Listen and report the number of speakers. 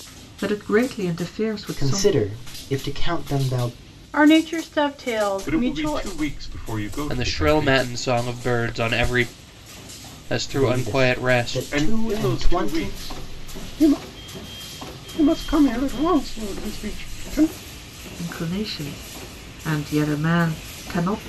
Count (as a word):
five